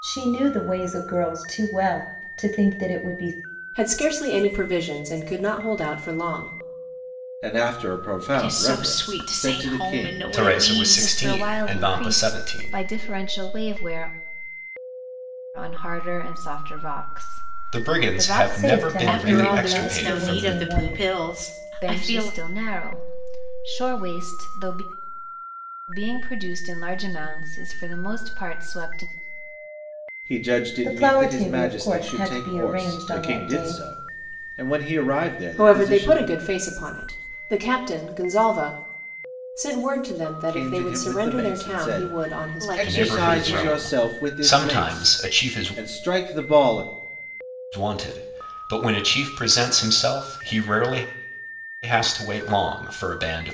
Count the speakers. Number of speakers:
six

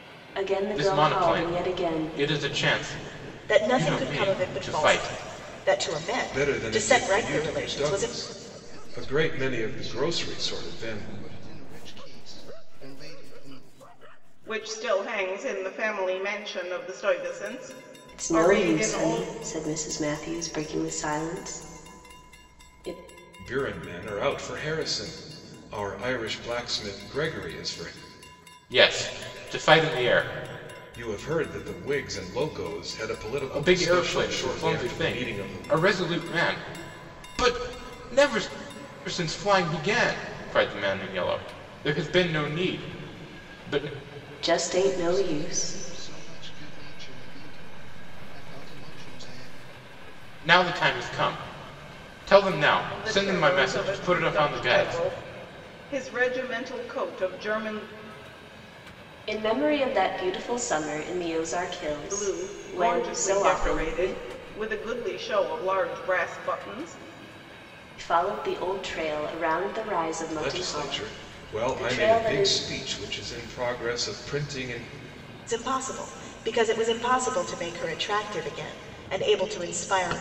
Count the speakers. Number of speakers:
six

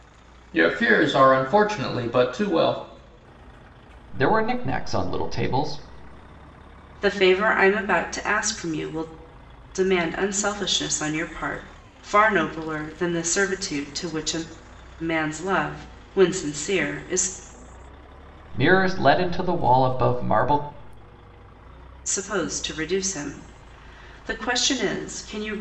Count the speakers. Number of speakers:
three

